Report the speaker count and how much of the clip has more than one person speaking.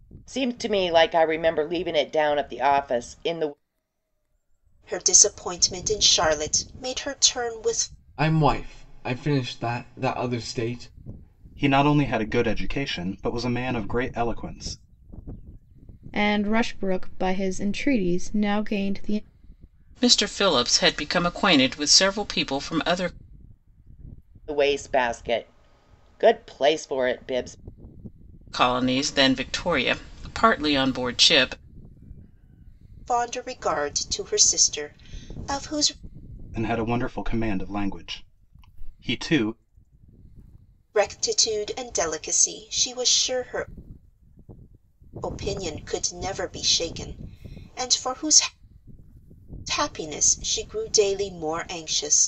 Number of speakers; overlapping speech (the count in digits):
6, no overlap